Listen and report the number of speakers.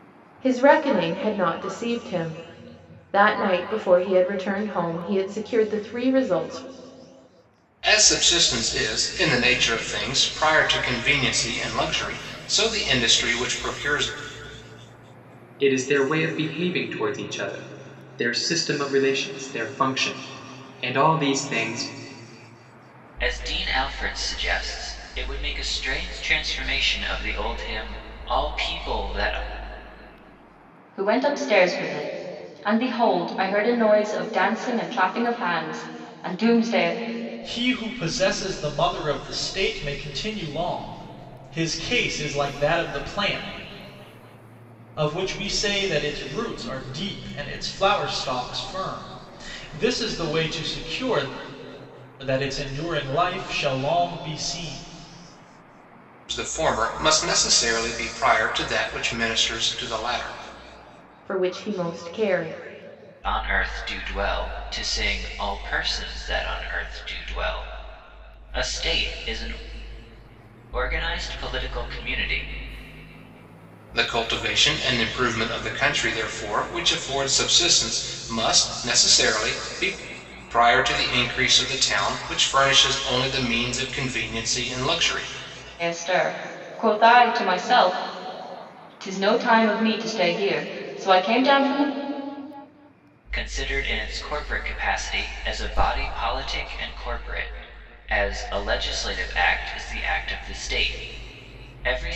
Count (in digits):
6